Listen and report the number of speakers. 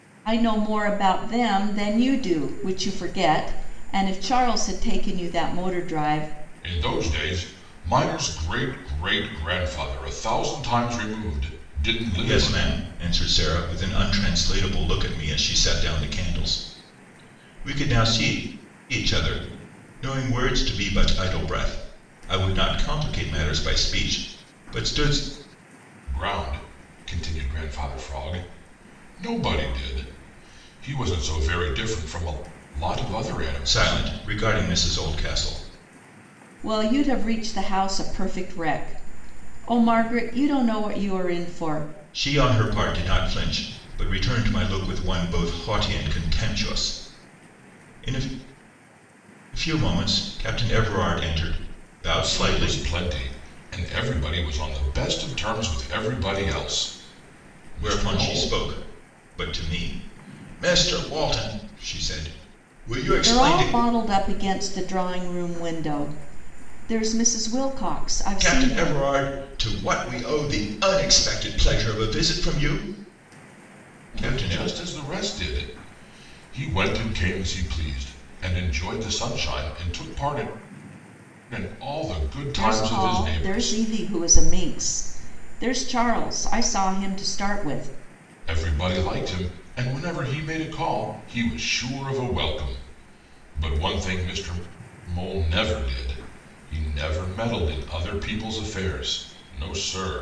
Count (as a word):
three